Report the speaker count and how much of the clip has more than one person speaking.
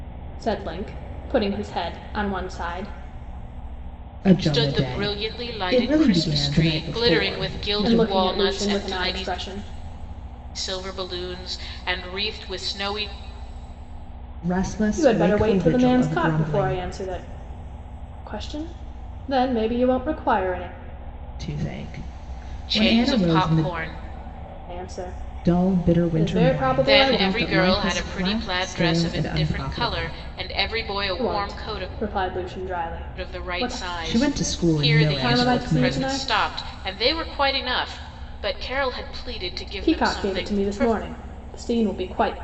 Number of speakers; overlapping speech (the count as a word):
three, about 40%